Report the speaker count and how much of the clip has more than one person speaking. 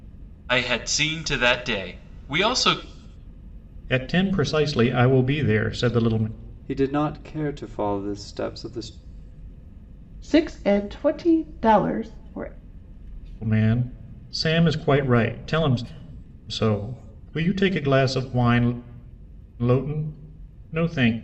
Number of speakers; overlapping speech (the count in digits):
4, no overlap